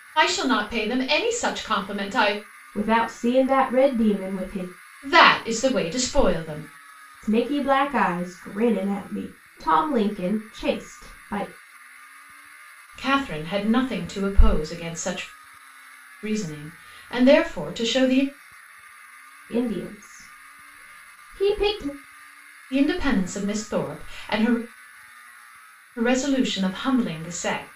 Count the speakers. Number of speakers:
two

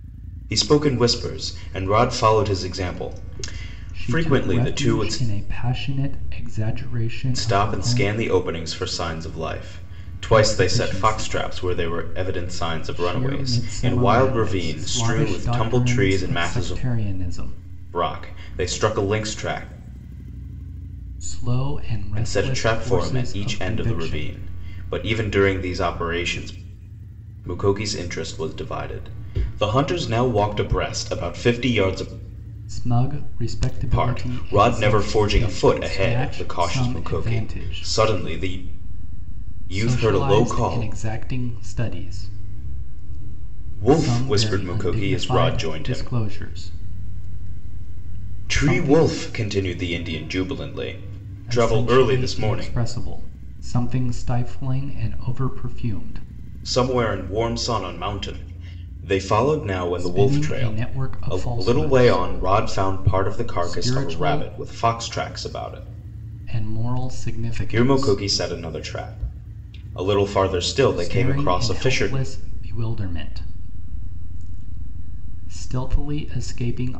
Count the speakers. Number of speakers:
two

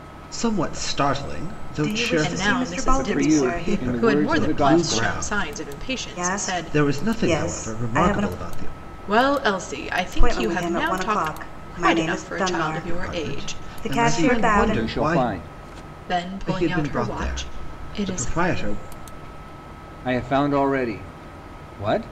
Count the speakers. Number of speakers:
four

